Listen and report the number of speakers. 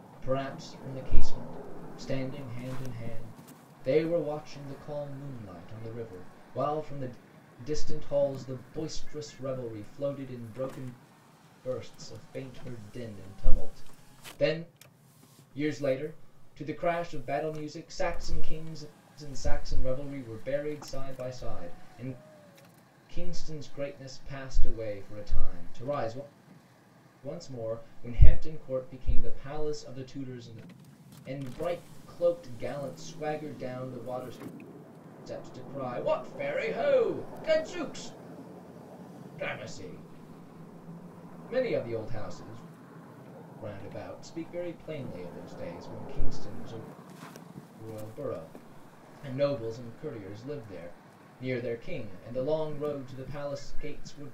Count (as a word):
one